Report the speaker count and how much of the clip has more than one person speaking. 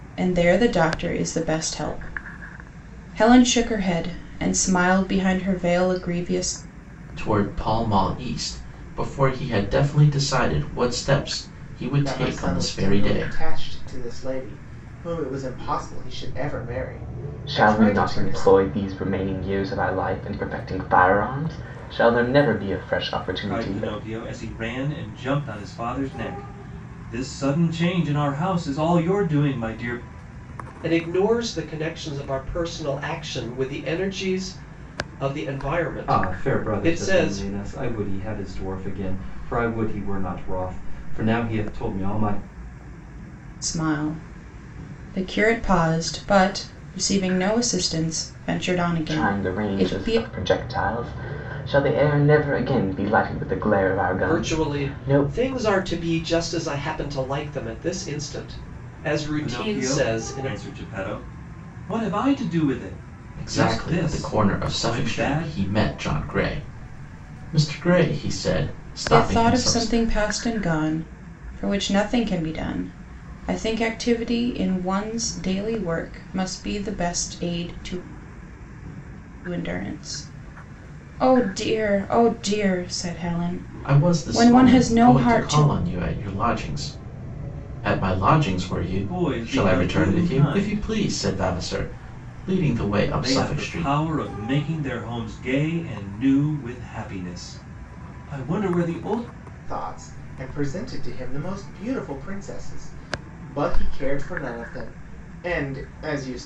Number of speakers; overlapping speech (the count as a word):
seven, about 15%